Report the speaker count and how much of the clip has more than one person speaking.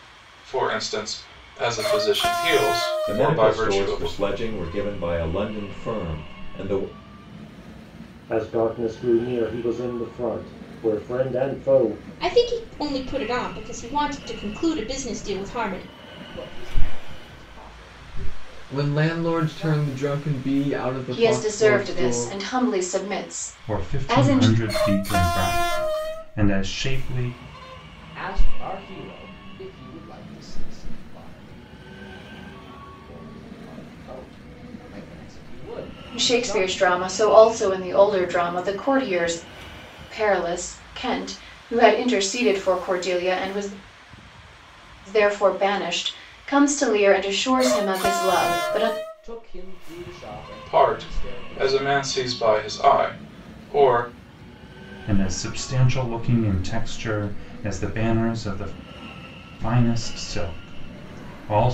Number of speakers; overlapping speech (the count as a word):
eight, about 12%